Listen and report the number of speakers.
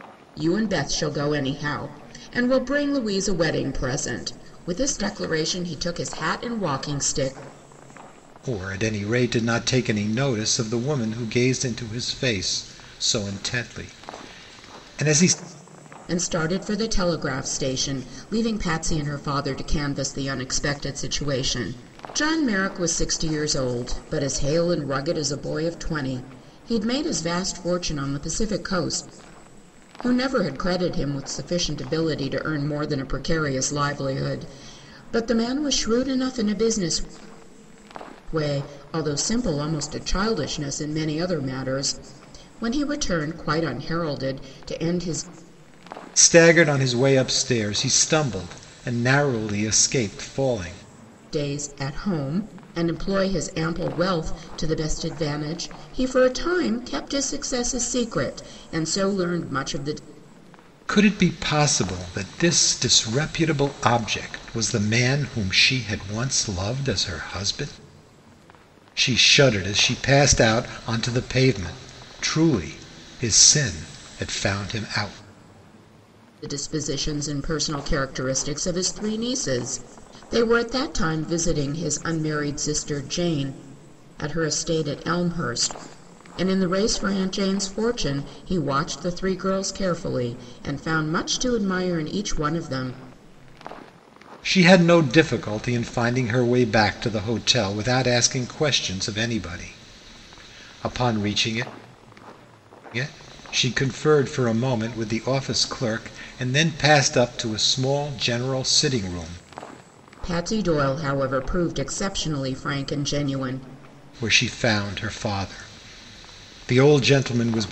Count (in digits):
2